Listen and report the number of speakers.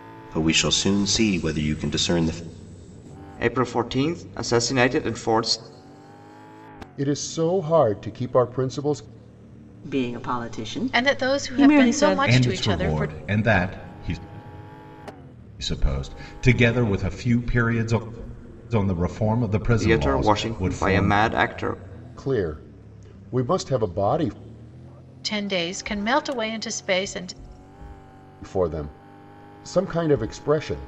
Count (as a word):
six